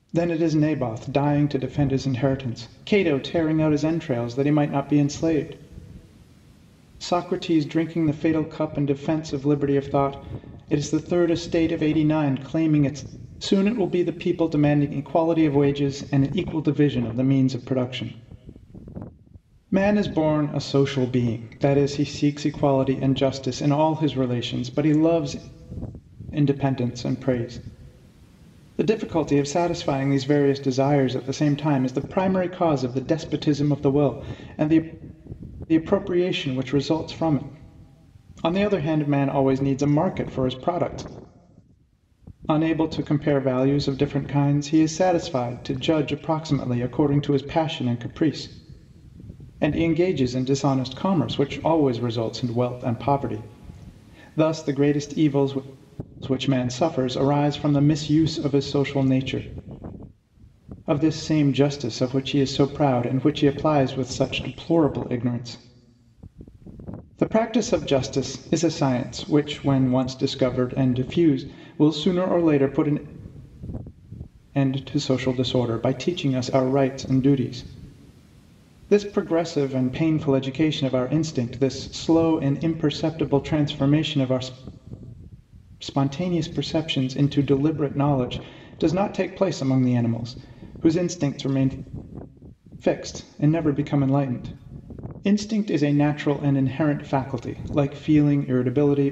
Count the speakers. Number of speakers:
1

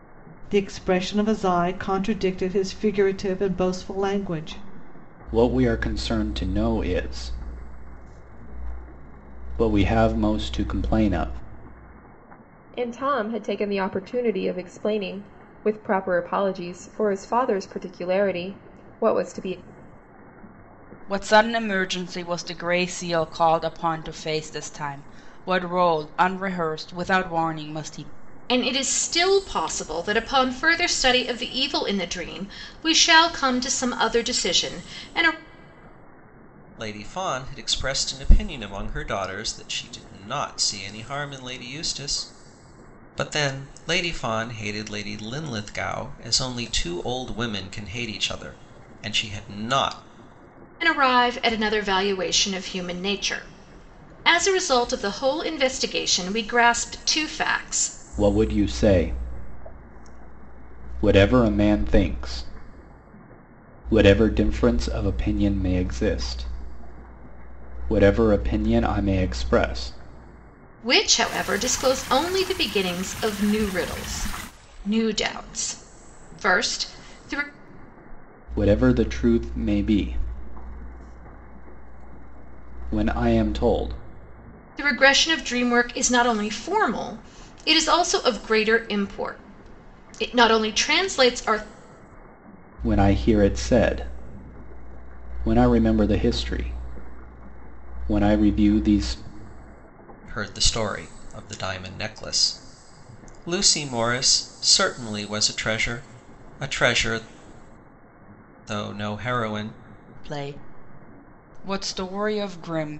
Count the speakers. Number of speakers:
6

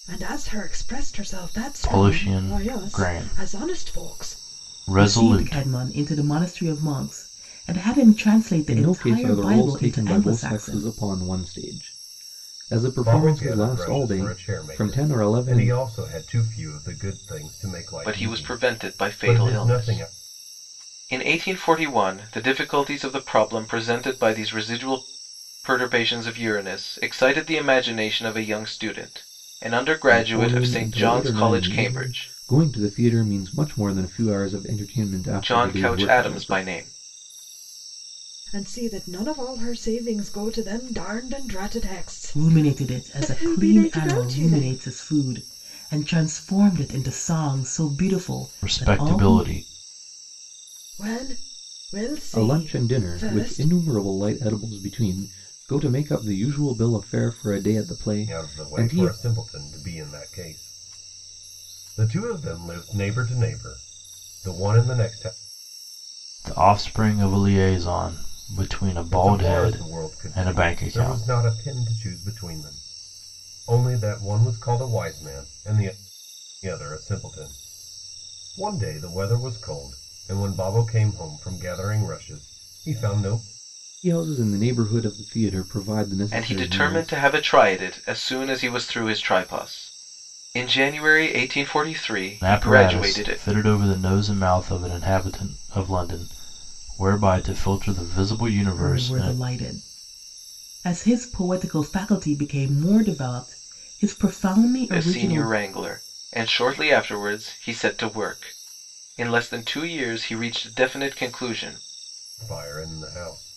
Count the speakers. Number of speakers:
6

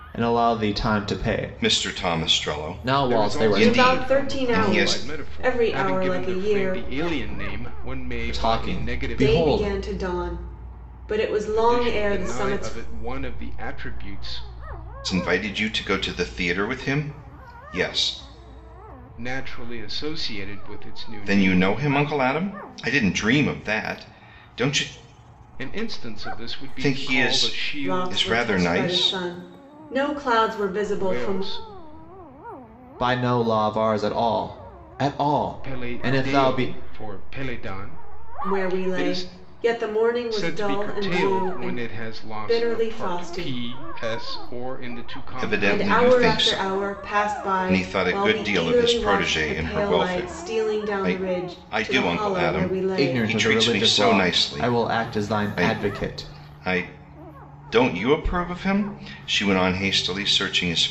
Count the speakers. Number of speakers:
4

